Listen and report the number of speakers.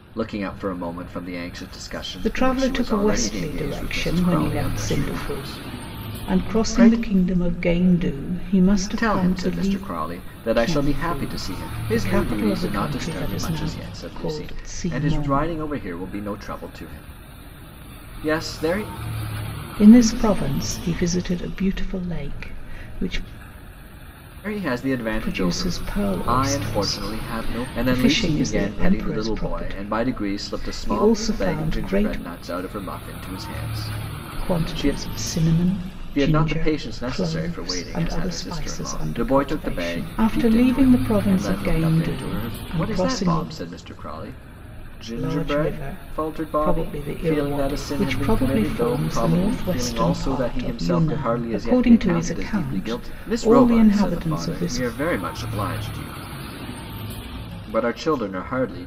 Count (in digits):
2